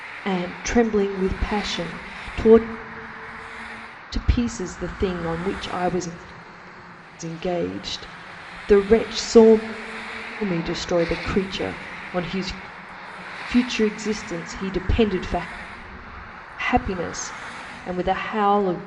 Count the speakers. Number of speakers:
one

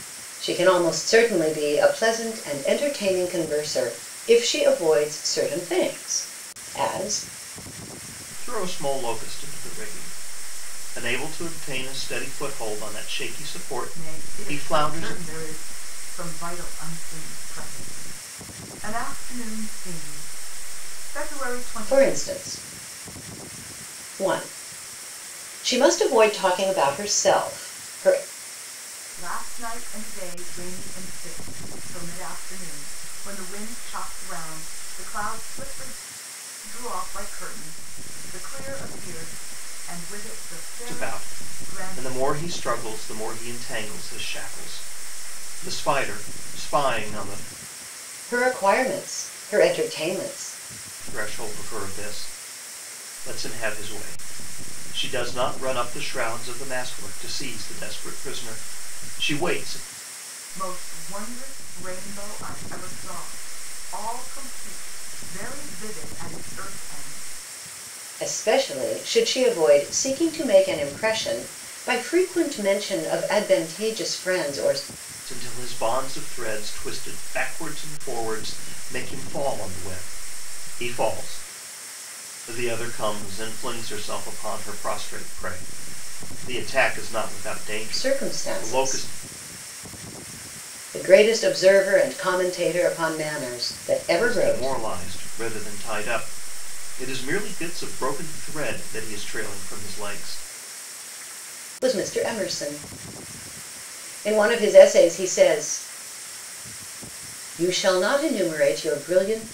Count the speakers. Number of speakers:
three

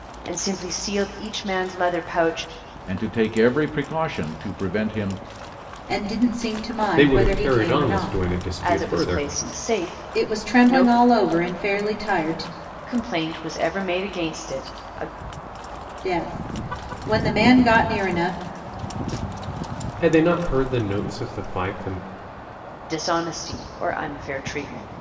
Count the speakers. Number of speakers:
four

